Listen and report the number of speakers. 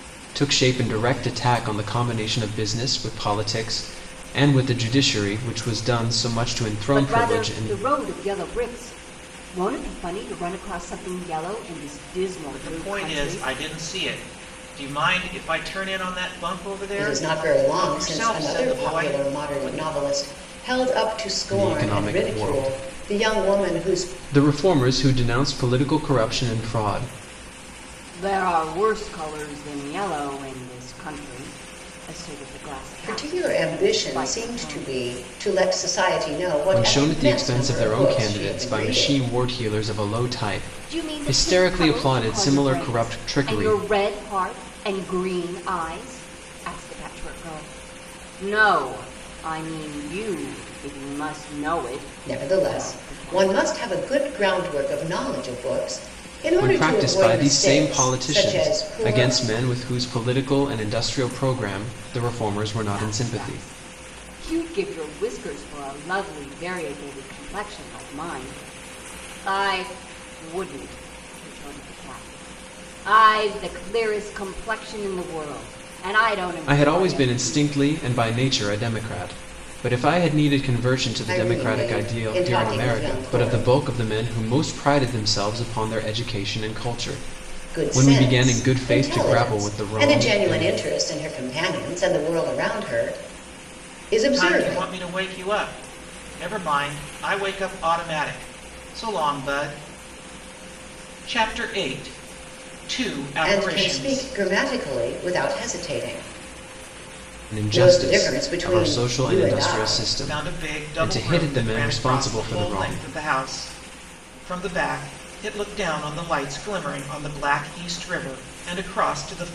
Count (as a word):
four